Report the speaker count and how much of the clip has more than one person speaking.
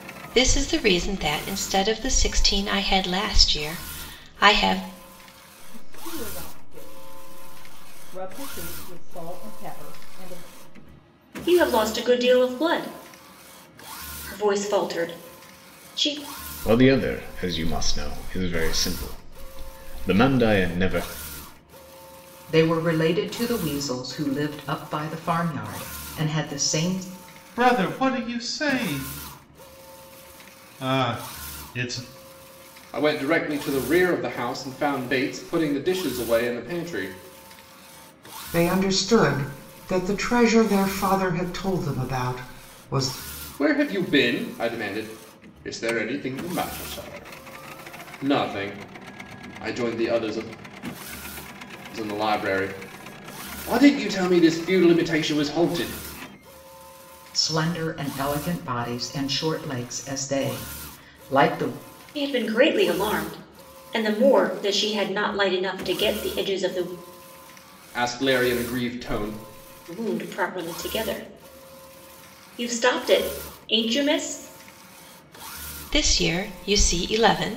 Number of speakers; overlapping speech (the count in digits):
8, no overlap